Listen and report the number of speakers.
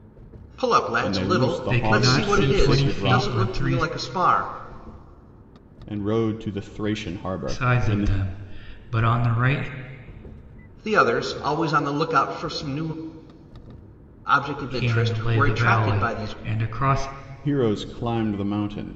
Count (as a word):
three